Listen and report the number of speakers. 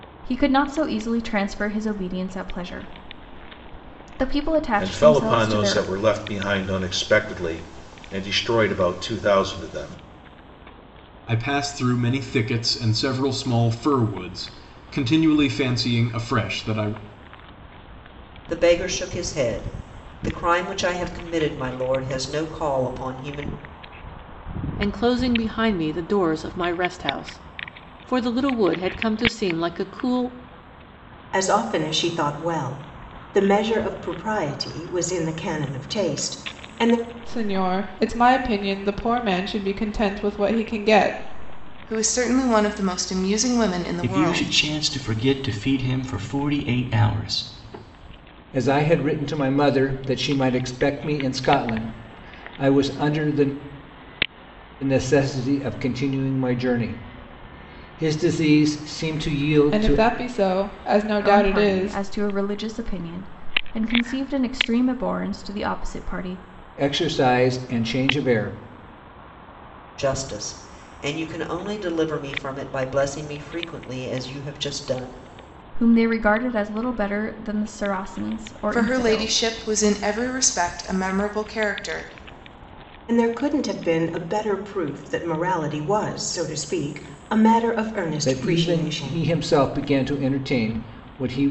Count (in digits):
10